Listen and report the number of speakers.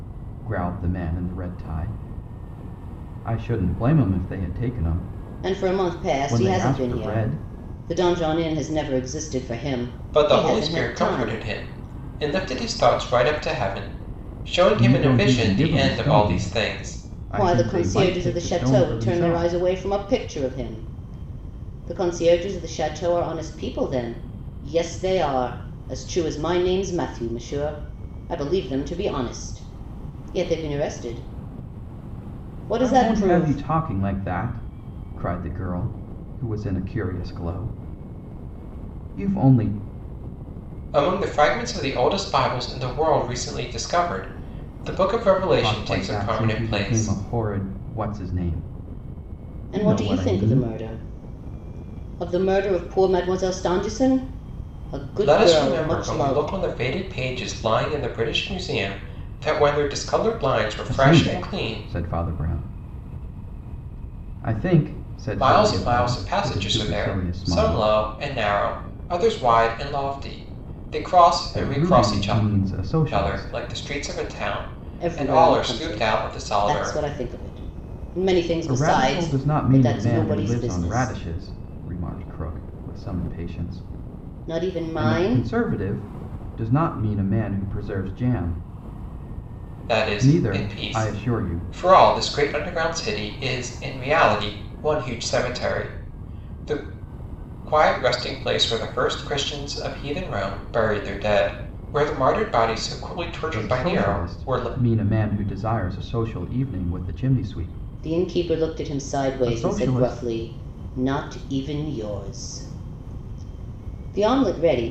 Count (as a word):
three